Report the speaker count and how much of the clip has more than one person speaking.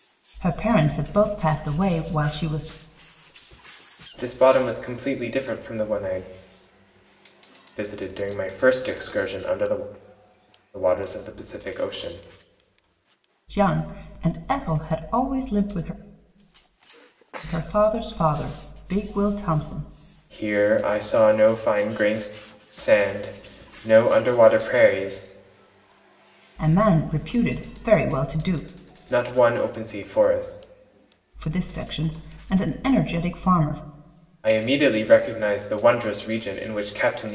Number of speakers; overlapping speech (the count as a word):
two, no overlap